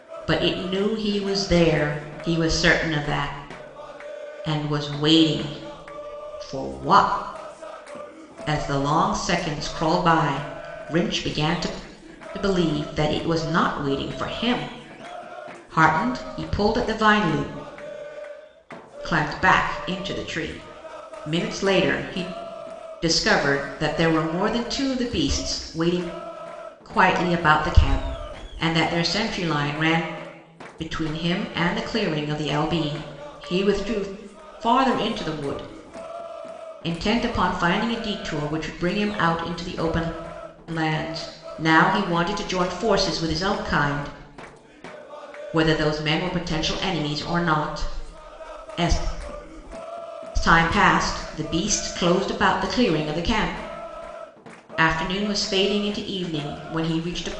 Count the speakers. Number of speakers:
one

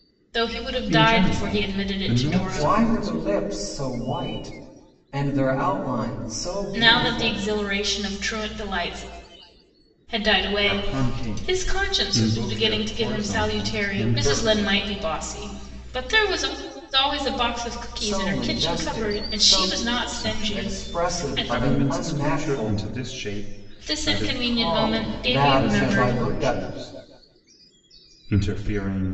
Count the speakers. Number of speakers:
three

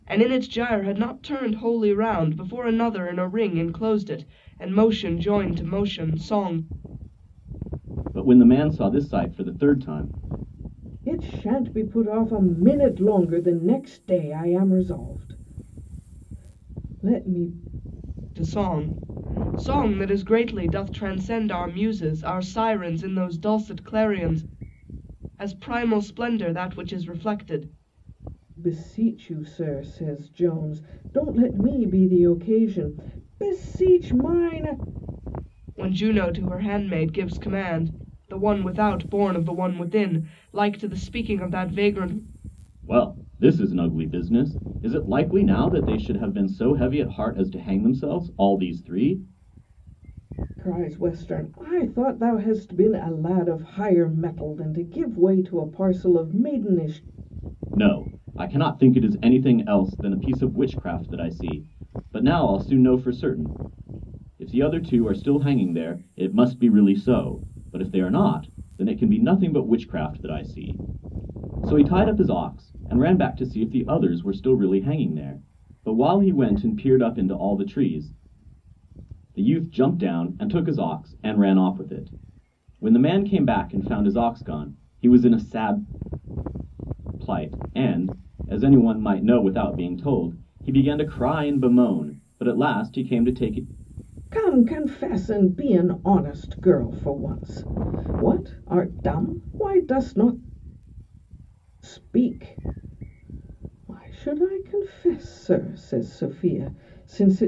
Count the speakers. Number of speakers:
three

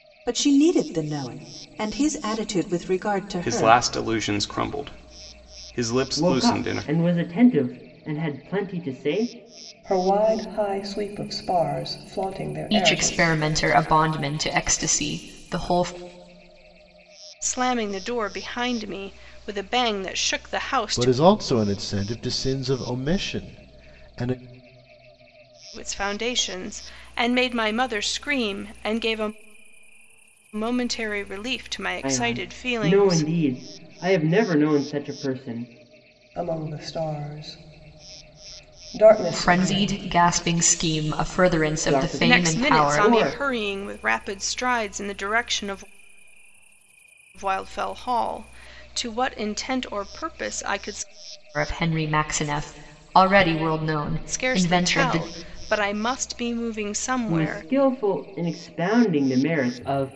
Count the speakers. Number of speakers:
seven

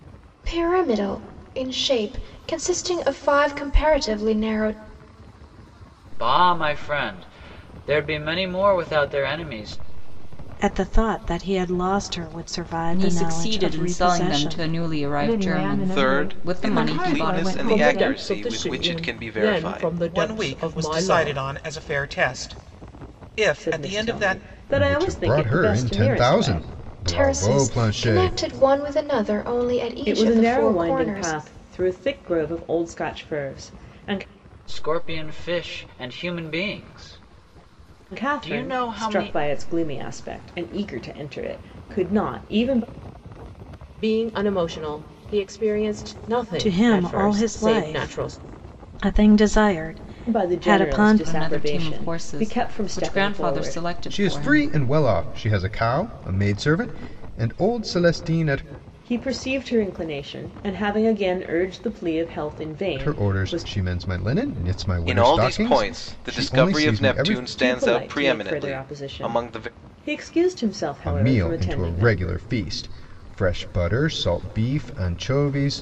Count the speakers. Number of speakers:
ten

